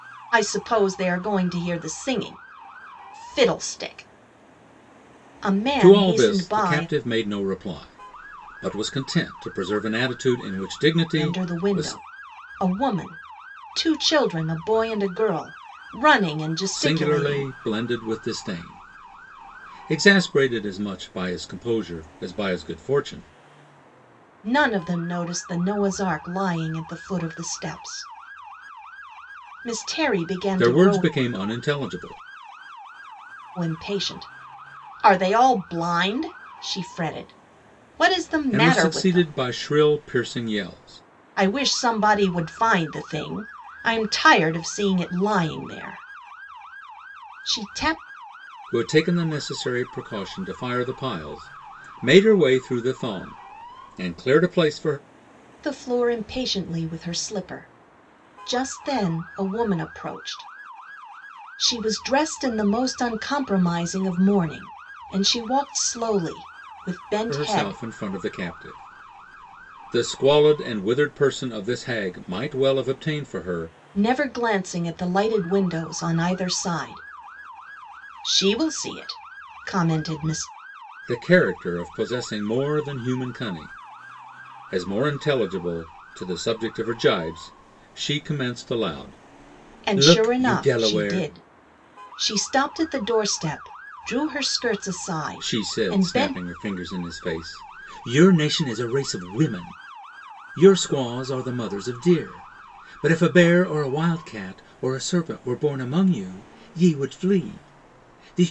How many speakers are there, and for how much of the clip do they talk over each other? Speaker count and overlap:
2, about 7%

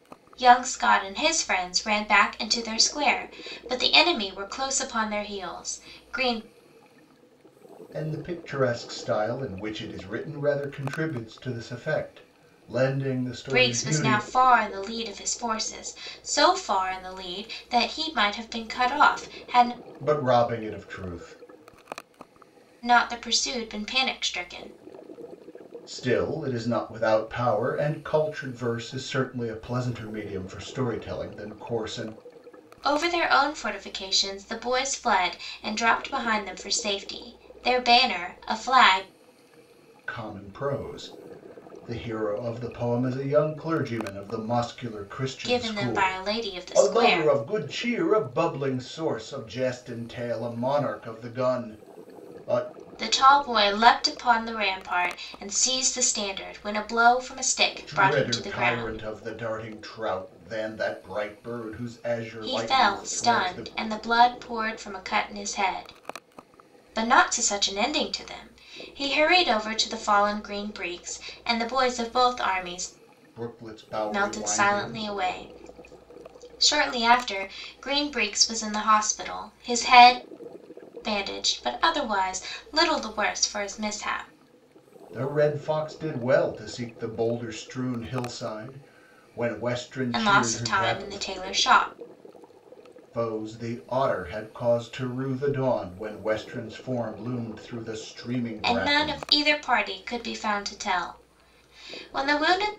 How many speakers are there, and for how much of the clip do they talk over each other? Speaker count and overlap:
2, about 8%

